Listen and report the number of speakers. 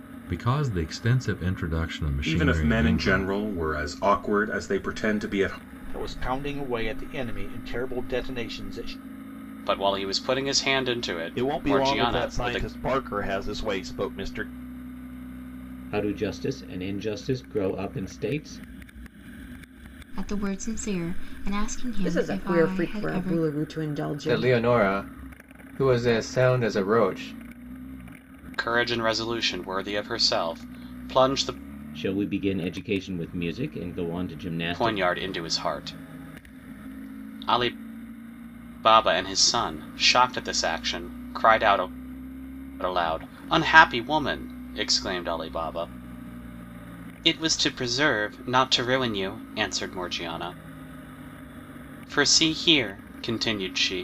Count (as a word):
nine